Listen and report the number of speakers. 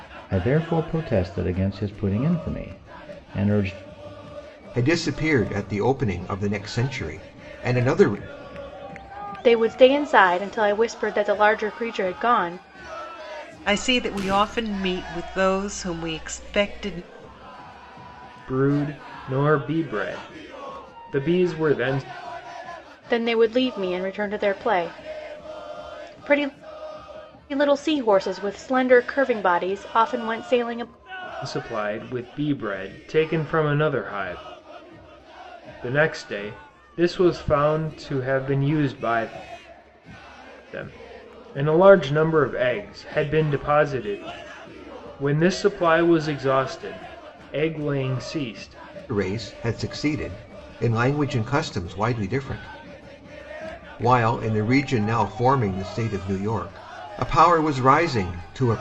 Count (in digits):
5